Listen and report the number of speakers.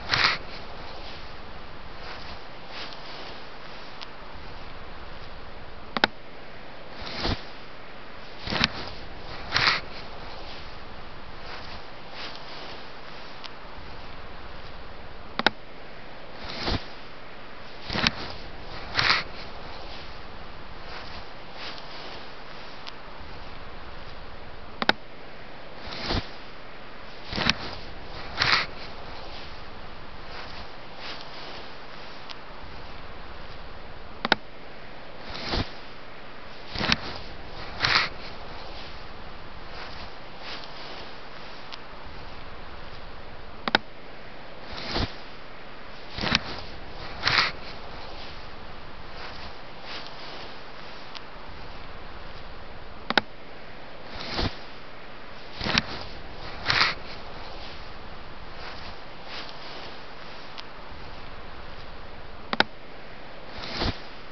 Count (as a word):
zero